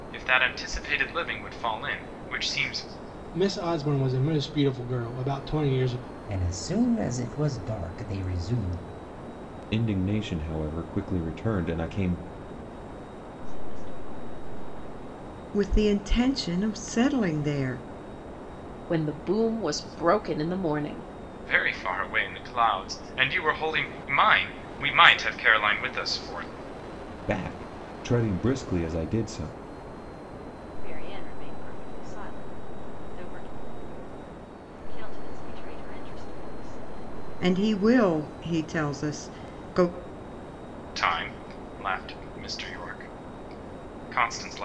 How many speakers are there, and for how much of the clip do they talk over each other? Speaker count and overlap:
7, no overlap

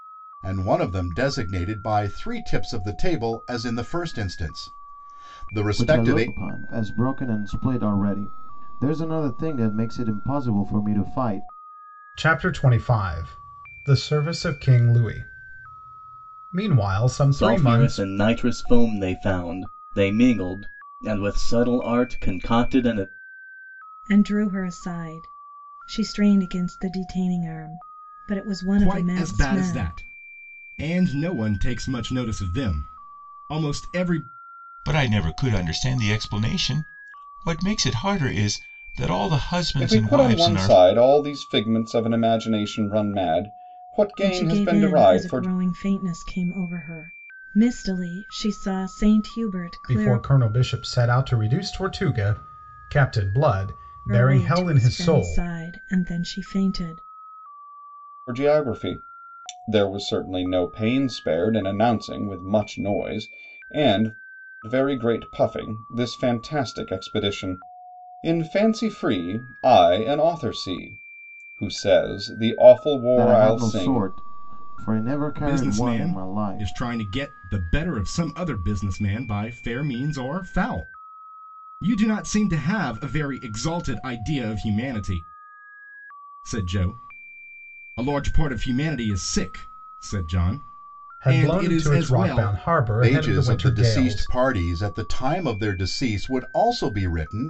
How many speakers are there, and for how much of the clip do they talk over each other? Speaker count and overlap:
8, about 12%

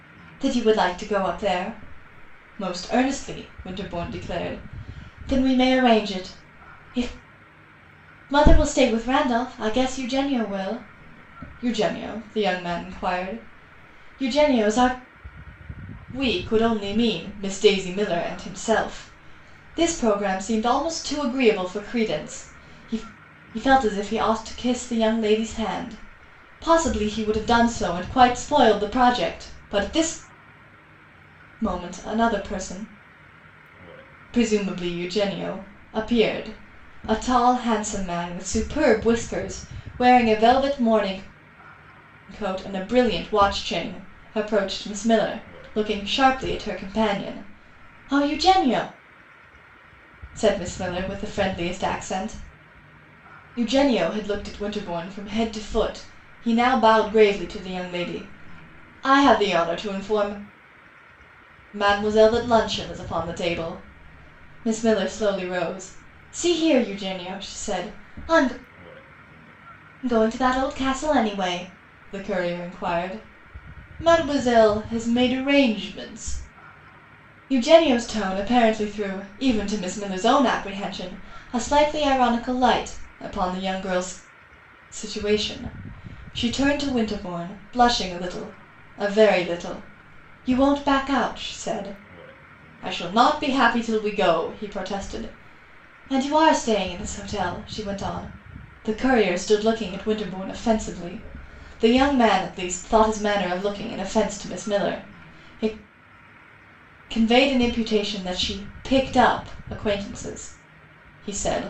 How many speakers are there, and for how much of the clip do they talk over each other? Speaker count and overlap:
1, no overlap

